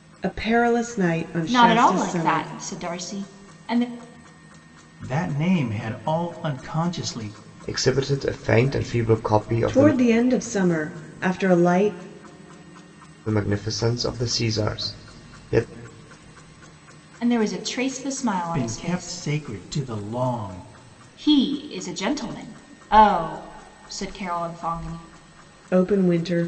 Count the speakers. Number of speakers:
four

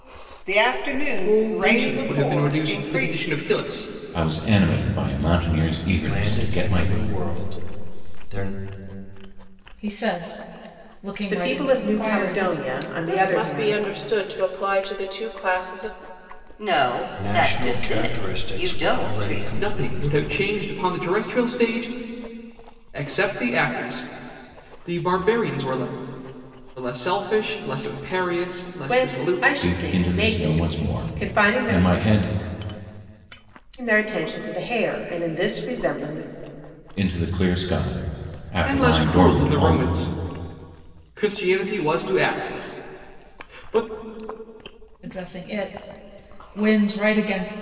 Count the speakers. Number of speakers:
eight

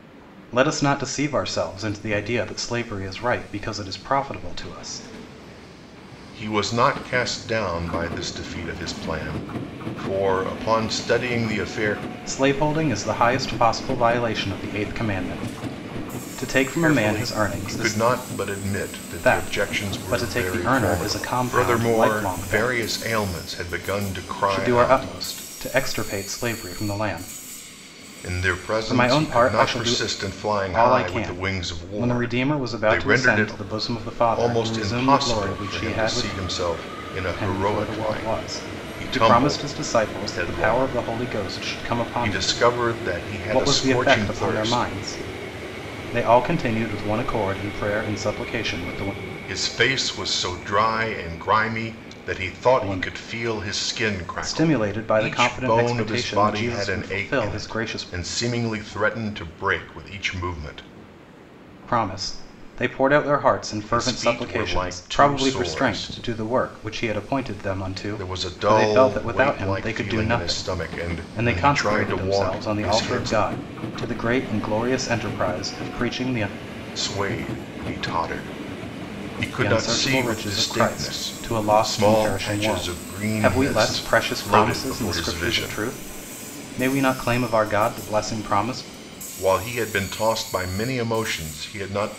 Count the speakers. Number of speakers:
two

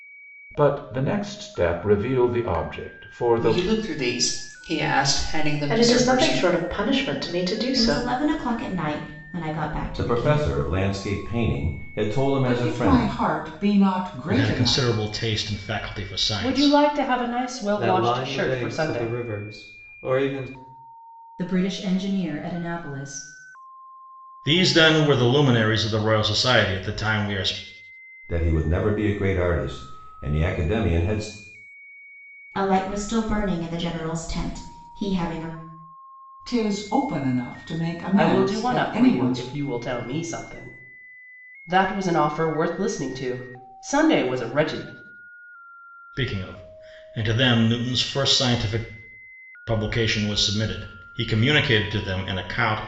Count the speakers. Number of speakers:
ten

